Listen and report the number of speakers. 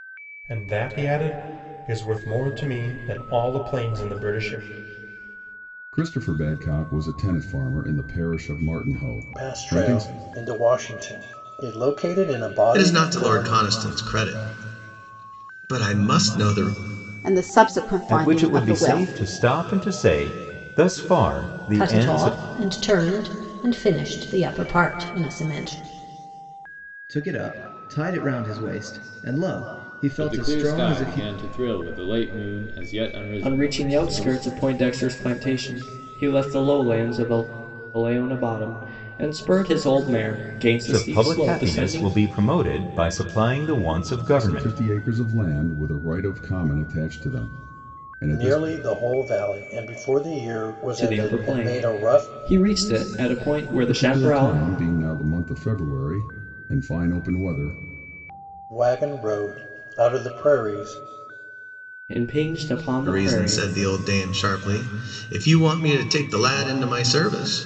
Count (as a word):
ten